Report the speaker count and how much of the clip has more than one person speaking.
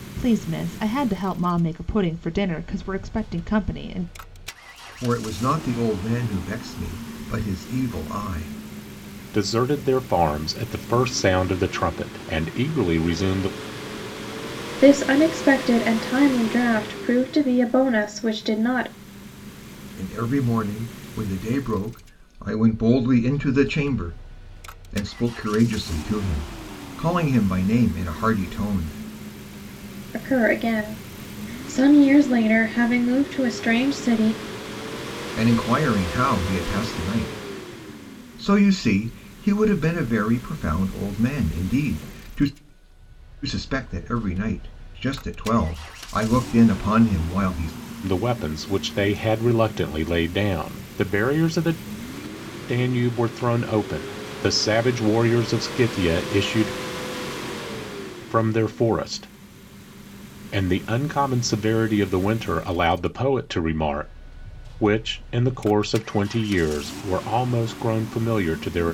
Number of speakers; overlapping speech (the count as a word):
four, no overlap